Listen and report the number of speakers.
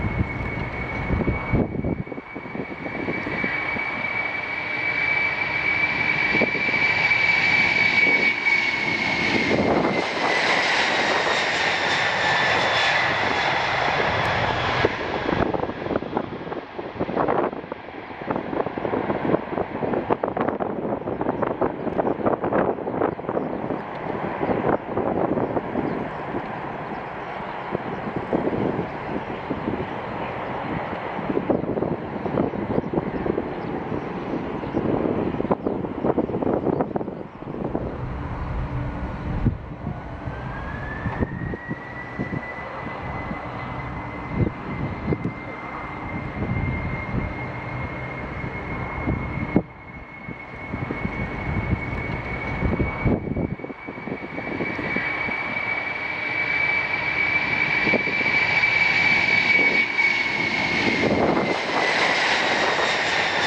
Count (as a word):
zero